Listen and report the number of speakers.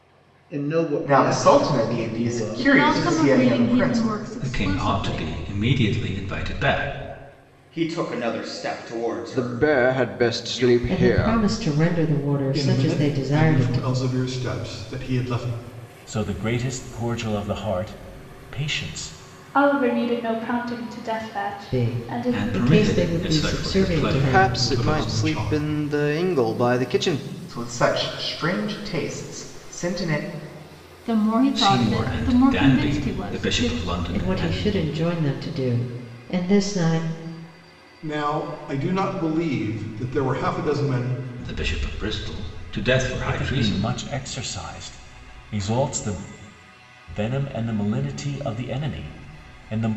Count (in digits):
10